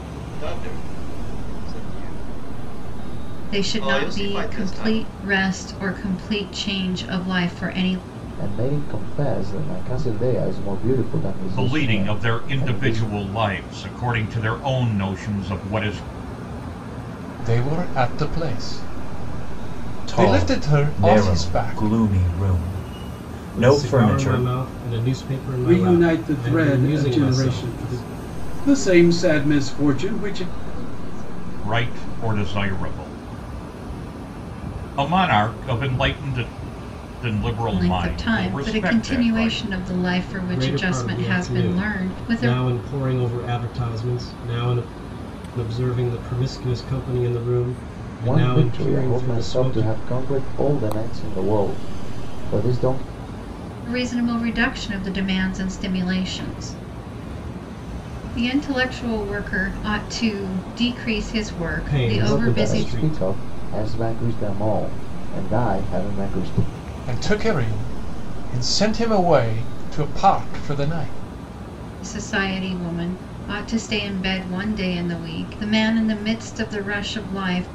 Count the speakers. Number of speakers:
9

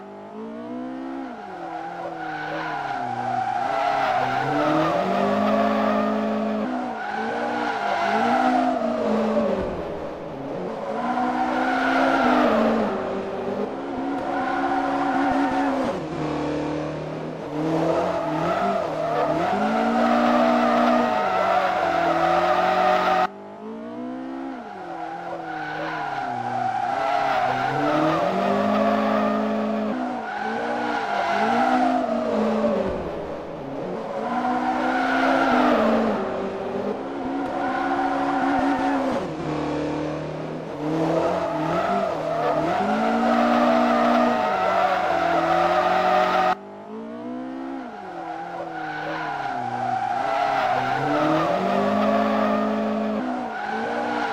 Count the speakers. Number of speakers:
0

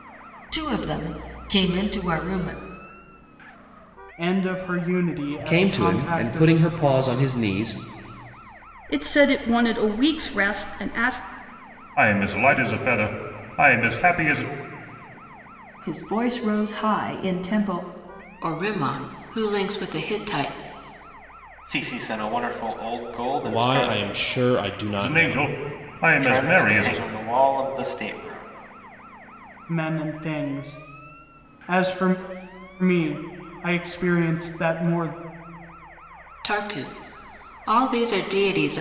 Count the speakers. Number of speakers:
9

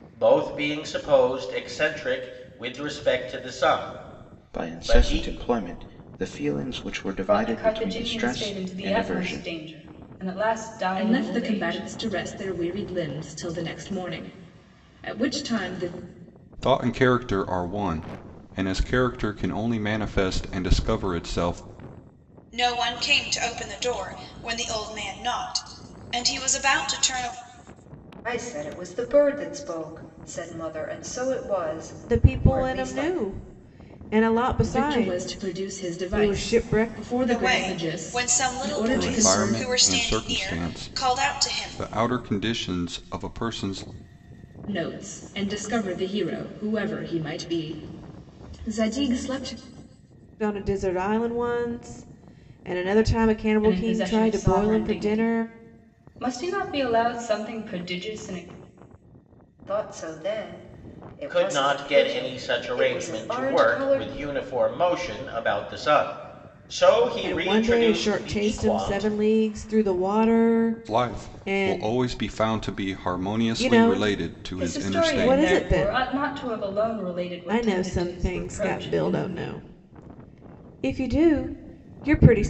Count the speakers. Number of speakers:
8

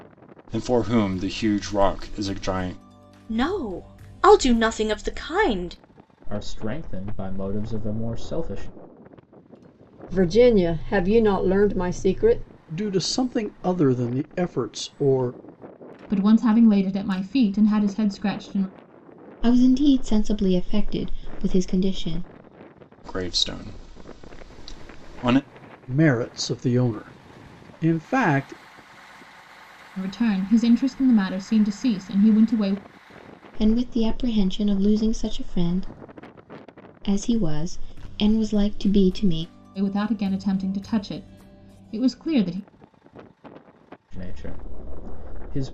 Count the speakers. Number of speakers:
7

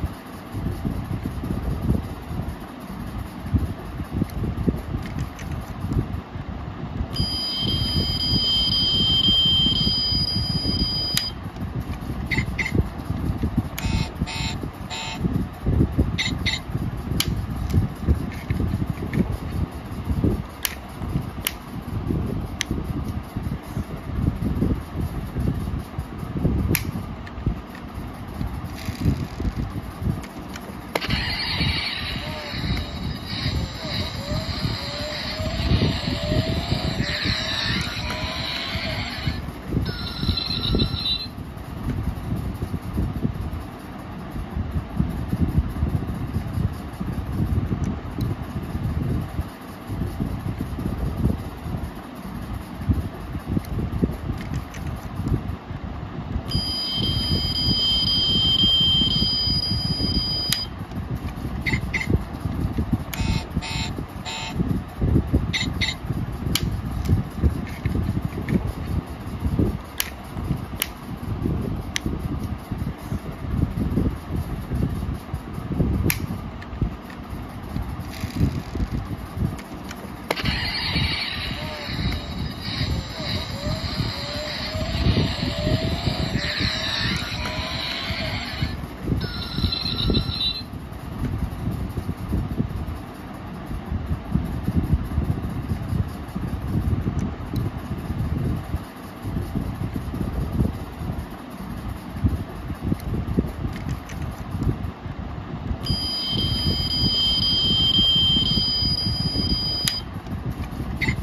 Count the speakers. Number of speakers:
0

